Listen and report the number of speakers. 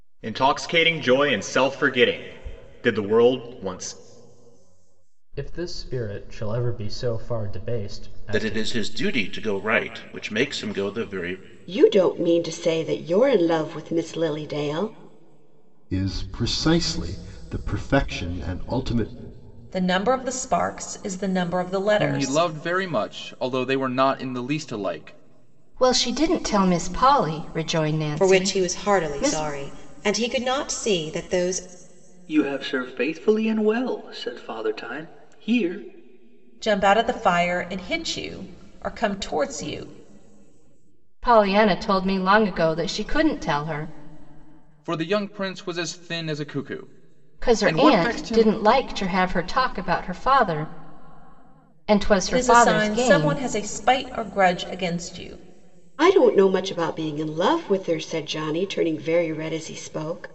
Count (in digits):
10